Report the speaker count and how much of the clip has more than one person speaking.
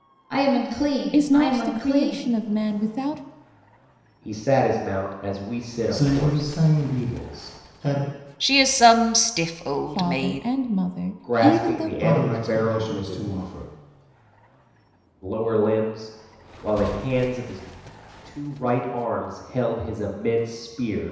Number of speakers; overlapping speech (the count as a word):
five, about 22%